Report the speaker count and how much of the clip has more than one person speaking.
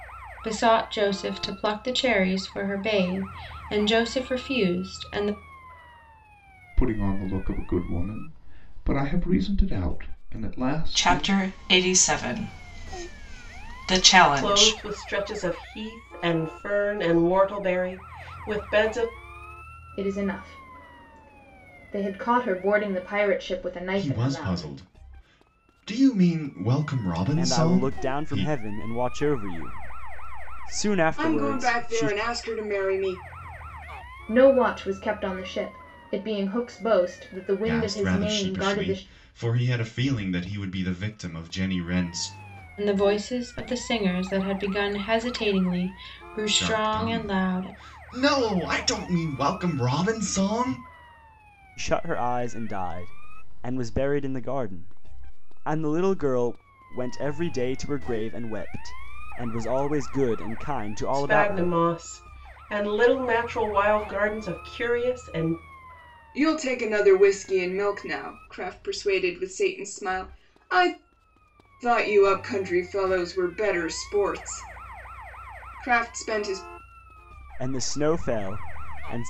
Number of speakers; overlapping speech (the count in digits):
8, about 9%